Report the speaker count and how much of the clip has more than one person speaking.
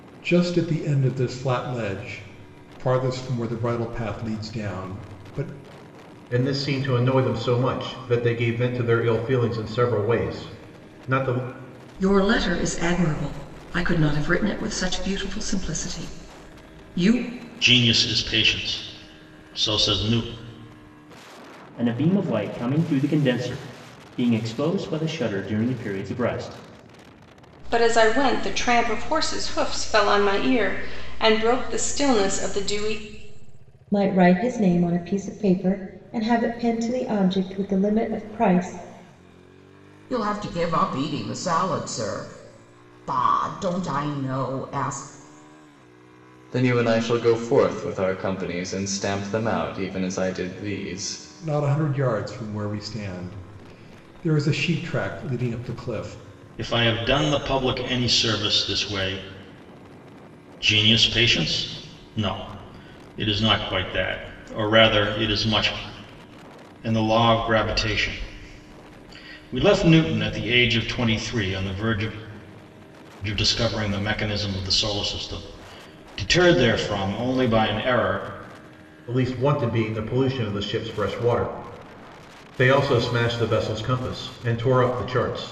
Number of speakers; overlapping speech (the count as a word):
nine, no overlap